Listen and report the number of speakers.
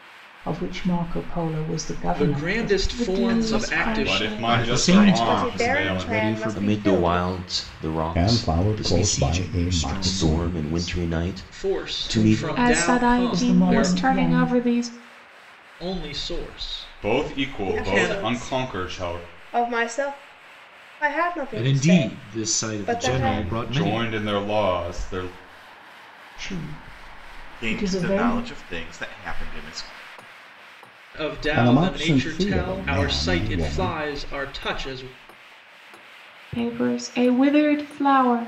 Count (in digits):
9